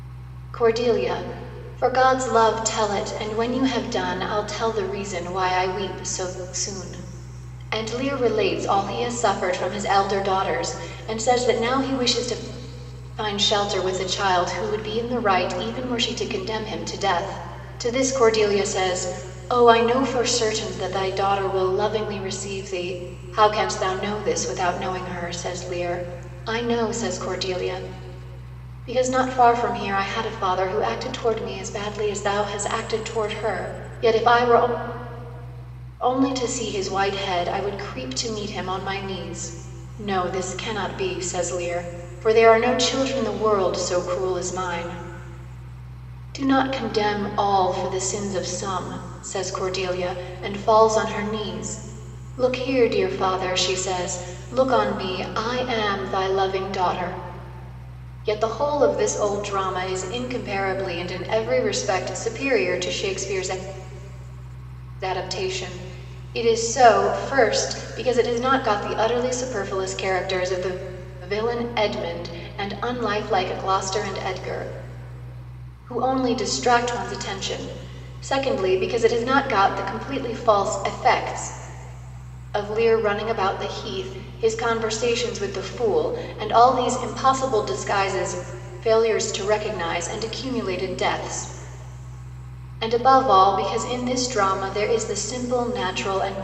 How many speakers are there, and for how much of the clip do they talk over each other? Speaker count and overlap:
1, no overlap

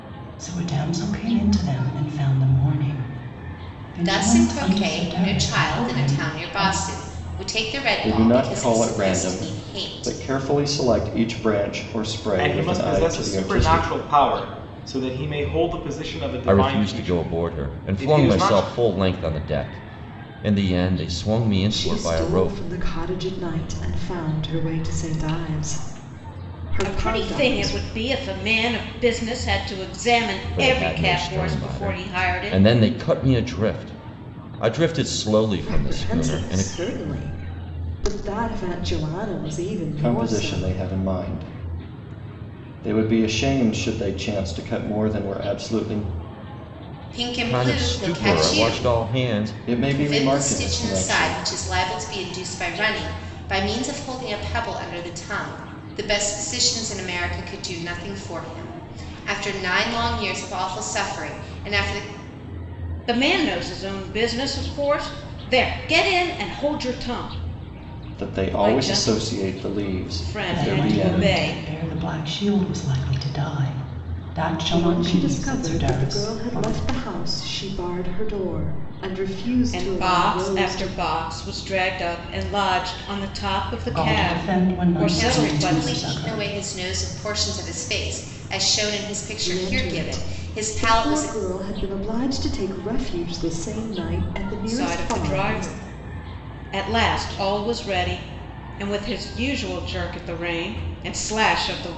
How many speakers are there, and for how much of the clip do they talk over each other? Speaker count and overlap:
7, about 29%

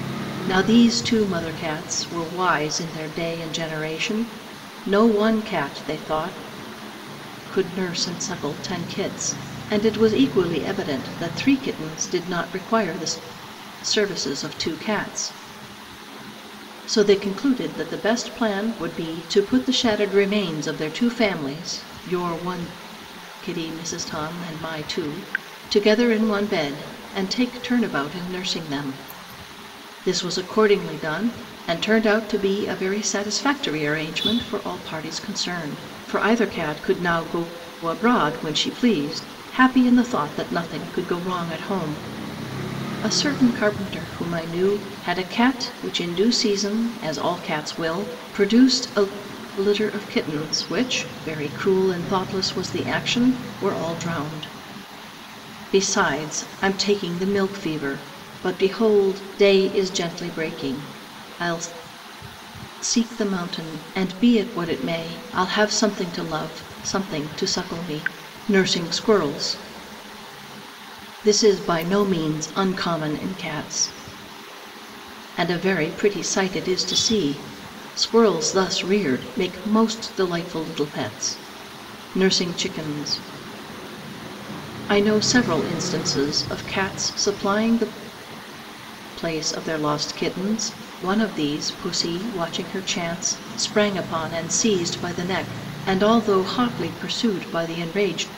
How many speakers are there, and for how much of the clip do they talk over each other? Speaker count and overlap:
1, no overlap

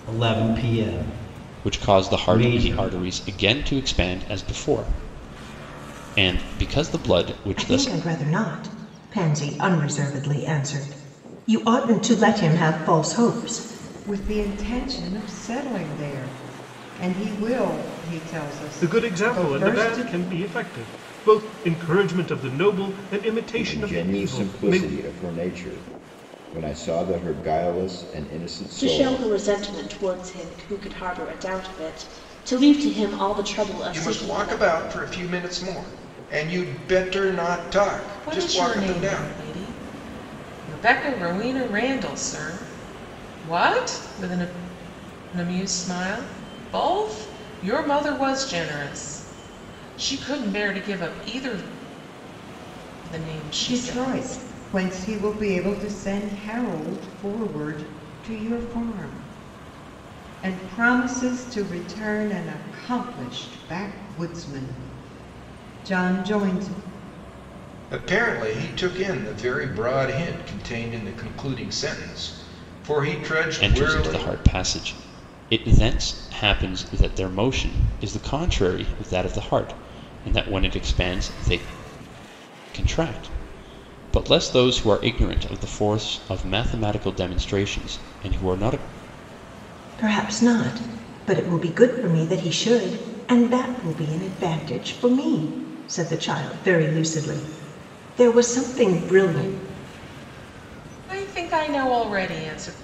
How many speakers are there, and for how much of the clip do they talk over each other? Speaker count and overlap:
9, about 8%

